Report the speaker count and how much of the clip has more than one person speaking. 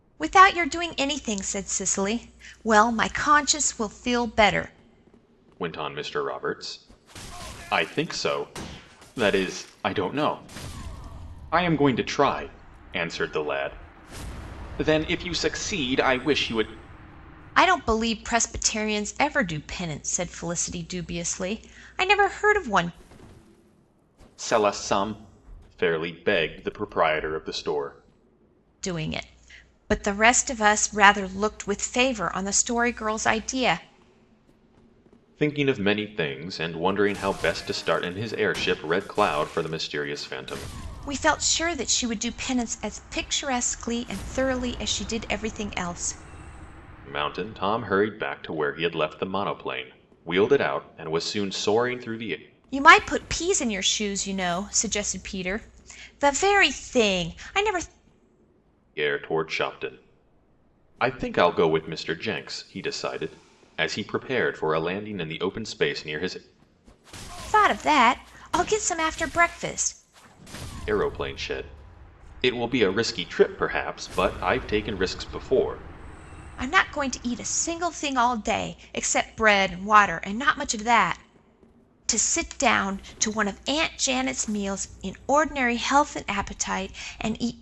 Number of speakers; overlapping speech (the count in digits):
2, no overlap